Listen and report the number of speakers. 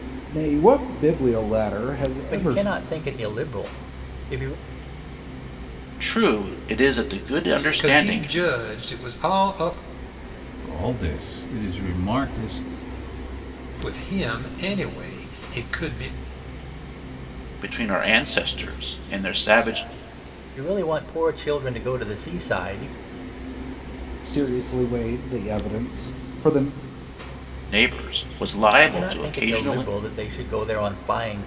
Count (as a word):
five